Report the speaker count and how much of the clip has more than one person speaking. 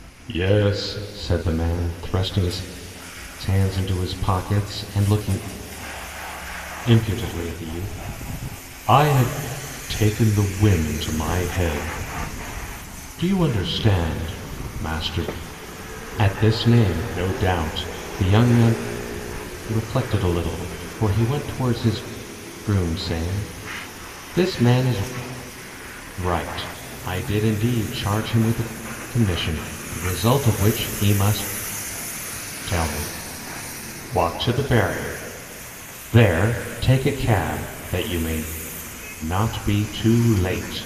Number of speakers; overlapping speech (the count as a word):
one, no overlap